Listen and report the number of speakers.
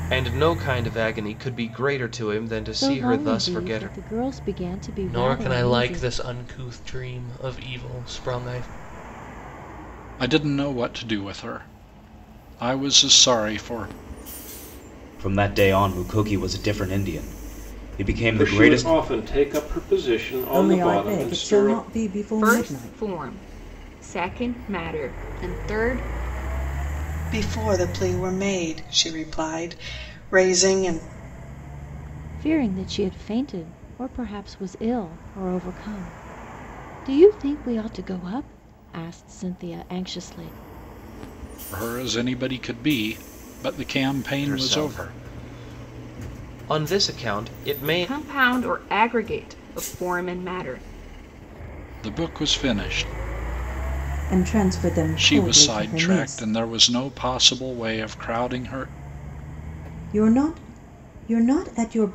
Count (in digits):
9